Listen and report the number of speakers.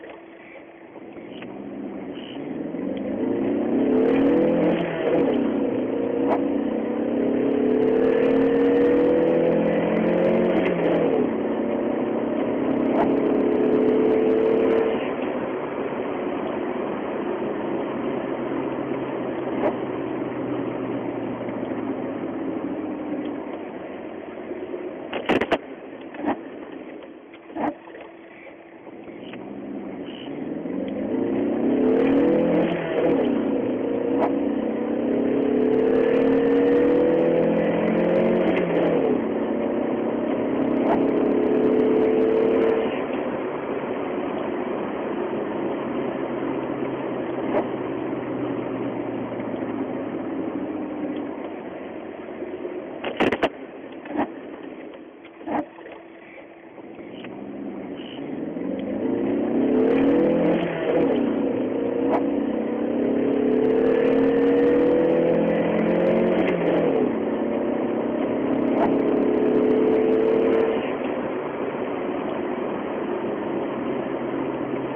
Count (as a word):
zero